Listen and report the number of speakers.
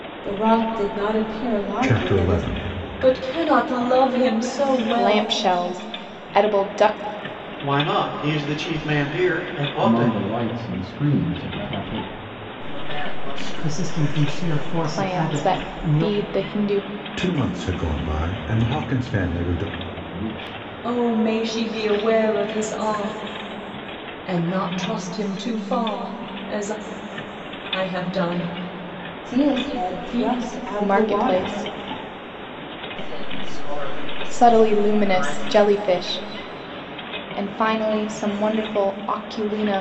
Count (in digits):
8